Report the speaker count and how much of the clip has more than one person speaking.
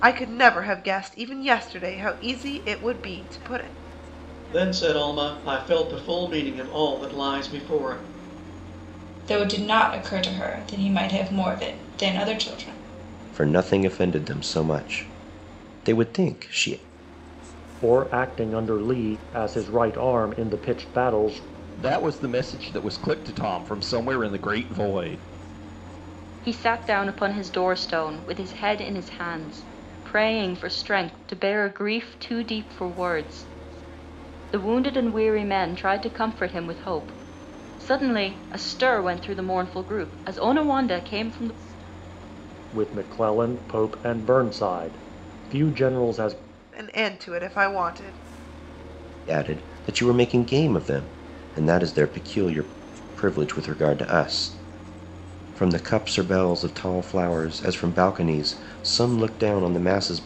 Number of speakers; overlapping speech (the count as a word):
seven, no overlap